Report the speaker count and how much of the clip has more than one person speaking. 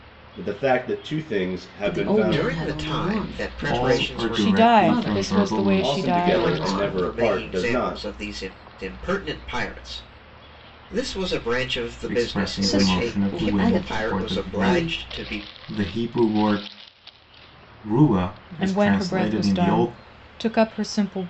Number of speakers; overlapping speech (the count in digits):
5, about 52%